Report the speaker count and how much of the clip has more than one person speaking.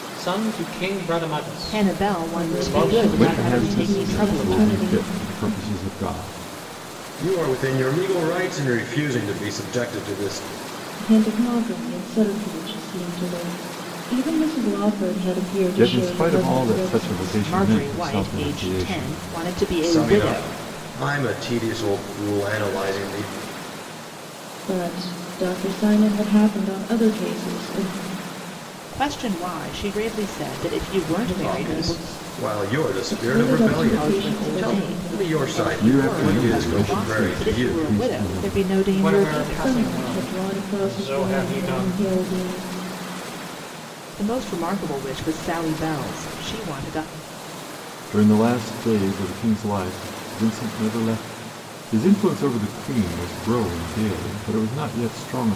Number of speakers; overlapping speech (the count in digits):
5, about 32%